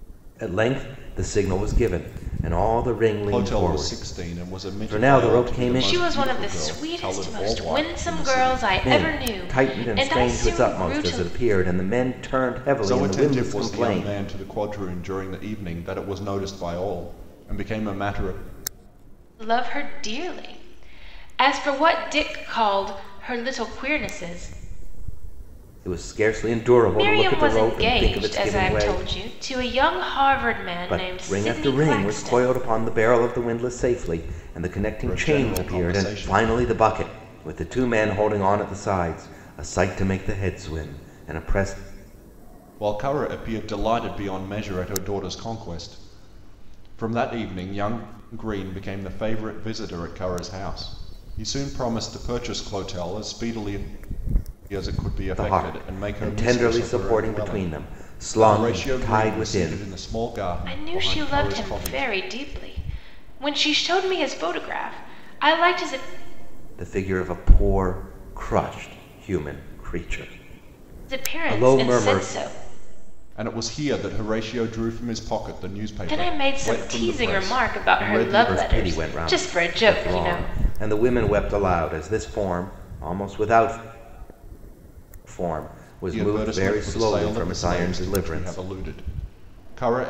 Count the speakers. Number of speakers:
3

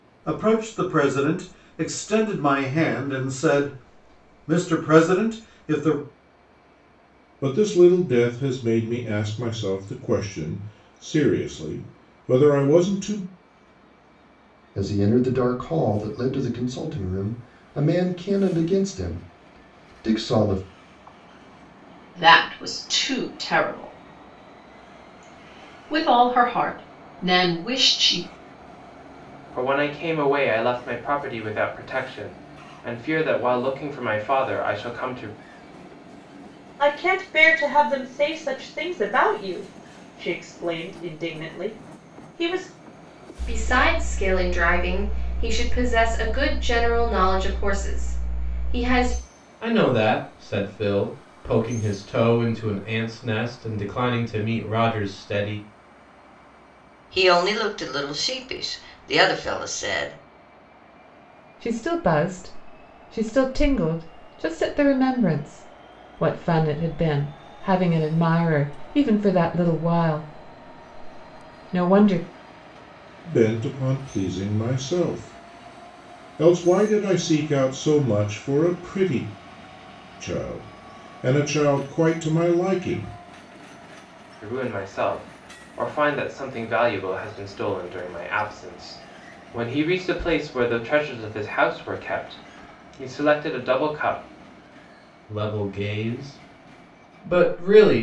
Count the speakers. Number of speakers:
10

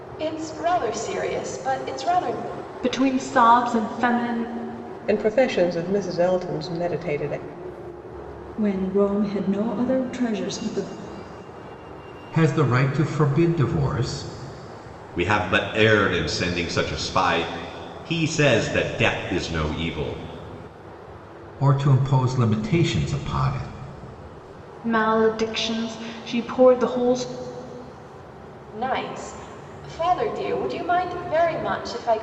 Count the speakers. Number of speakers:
6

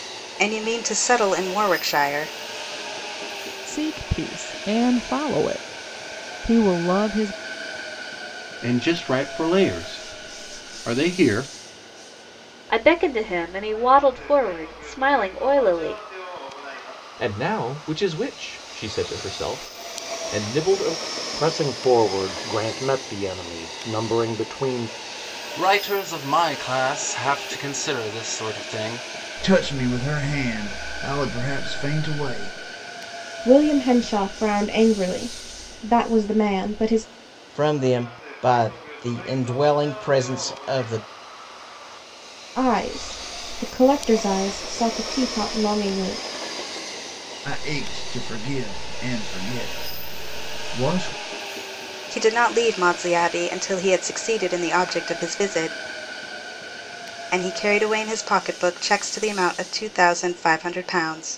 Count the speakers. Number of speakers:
10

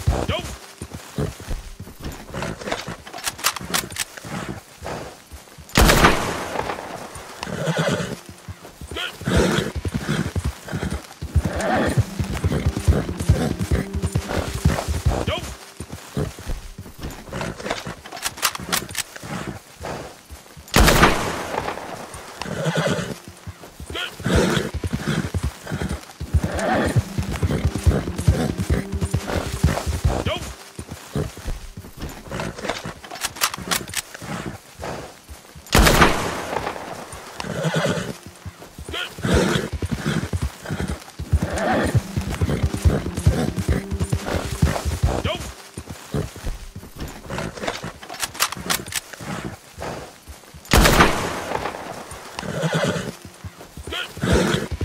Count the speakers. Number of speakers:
0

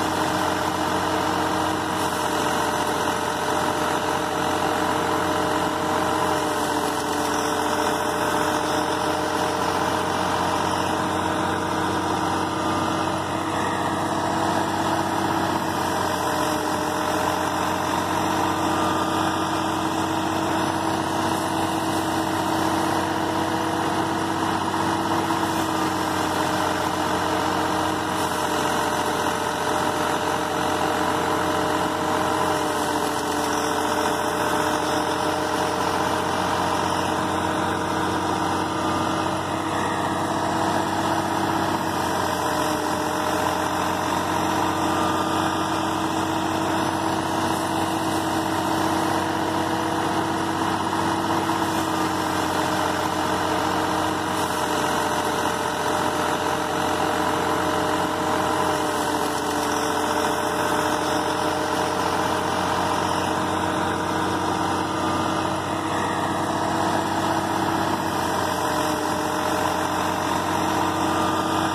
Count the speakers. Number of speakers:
0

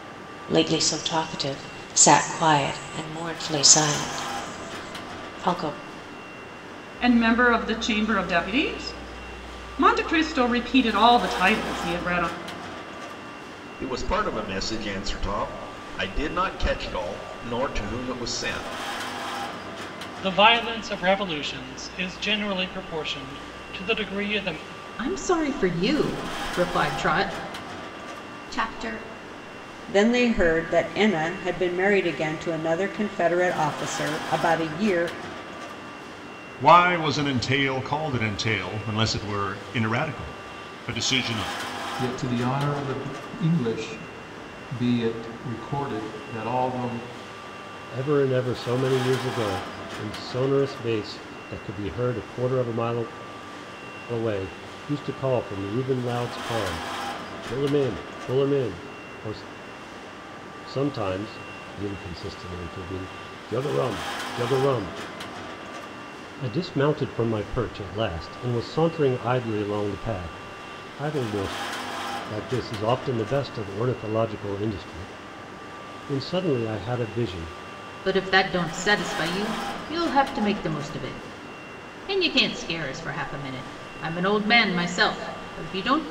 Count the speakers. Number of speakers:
10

